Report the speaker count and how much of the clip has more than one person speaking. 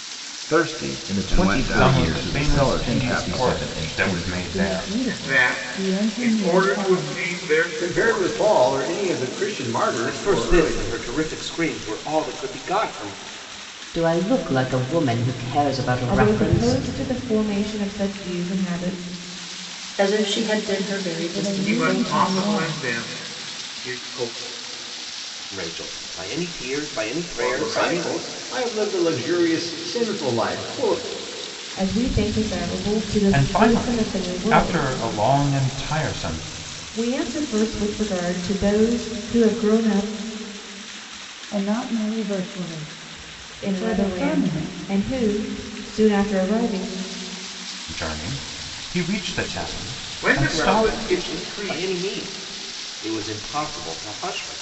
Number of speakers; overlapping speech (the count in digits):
10, about 28%